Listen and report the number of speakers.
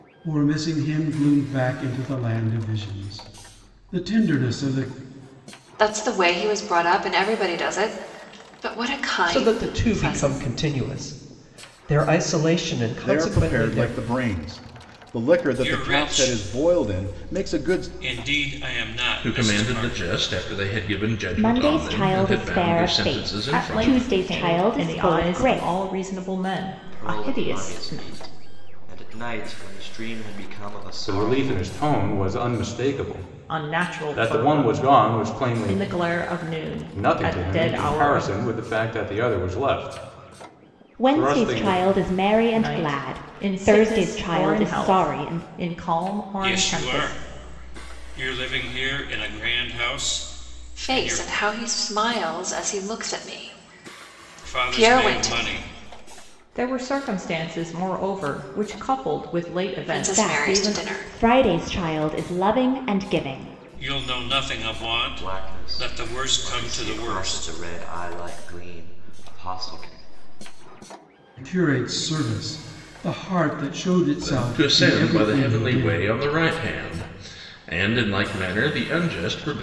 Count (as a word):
ten